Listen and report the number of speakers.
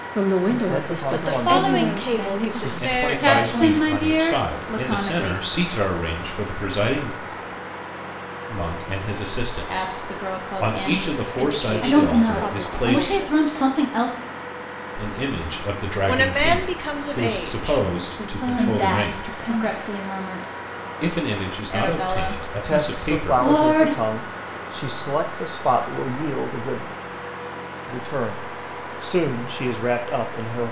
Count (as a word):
six